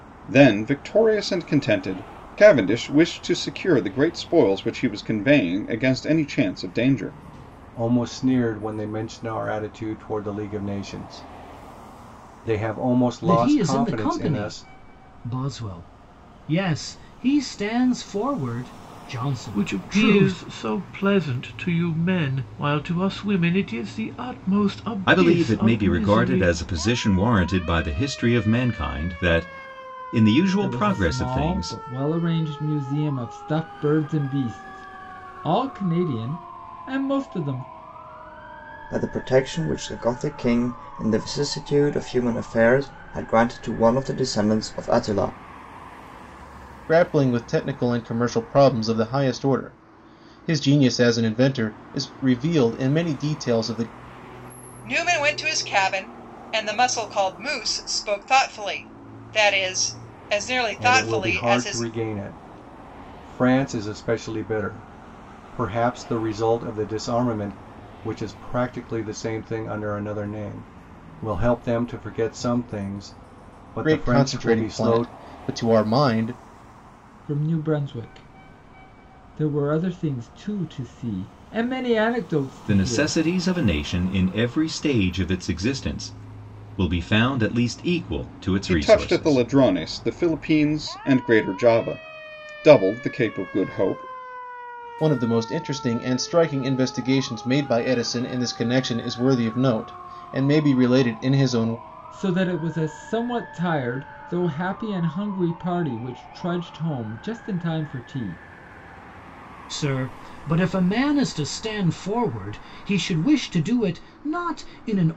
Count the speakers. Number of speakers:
9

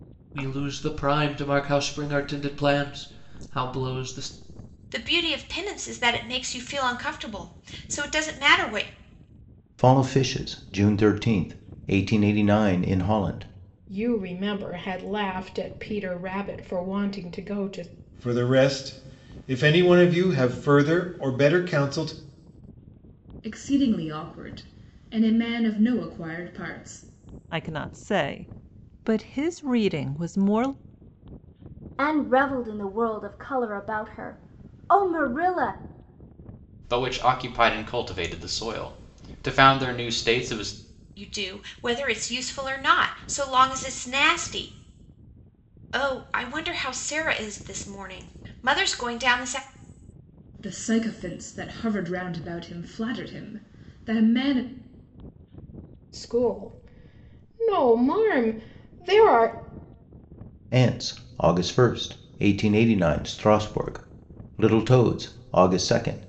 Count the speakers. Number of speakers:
9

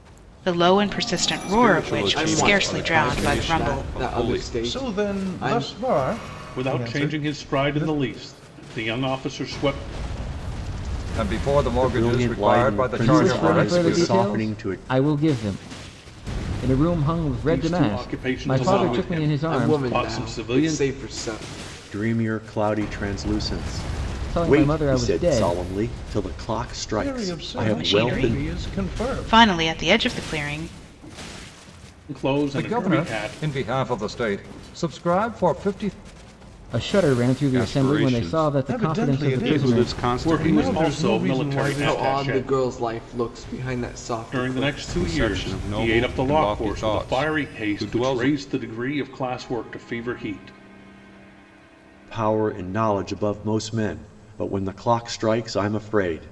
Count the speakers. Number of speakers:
8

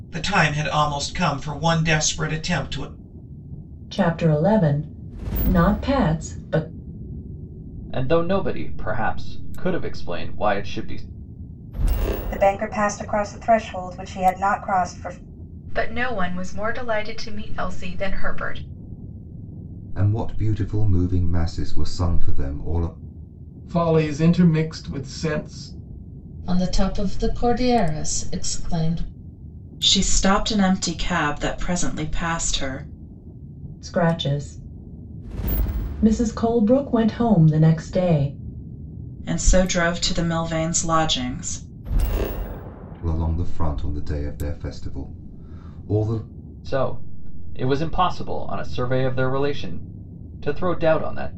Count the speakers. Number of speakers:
9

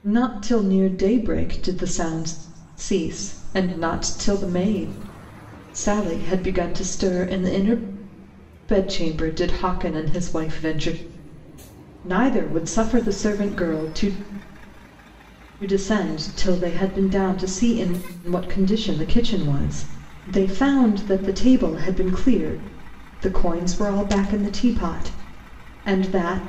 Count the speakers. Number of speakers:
1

